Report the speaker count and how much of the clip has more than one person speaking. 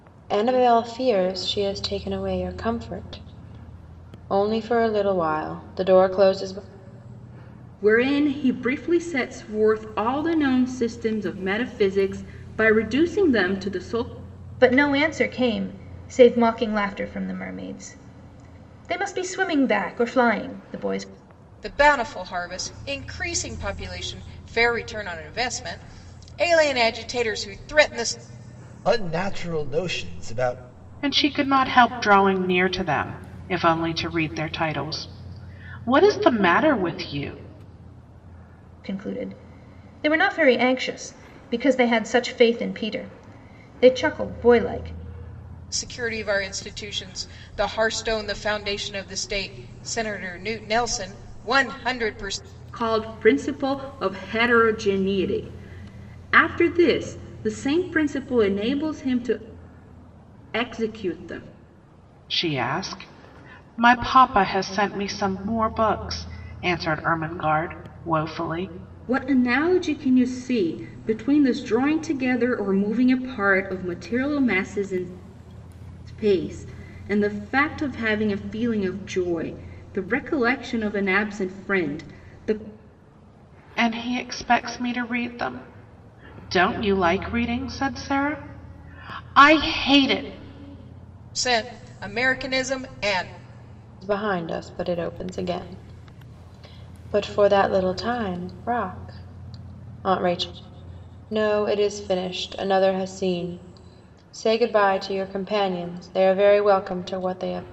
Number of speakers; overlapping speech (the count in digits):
6, no overlap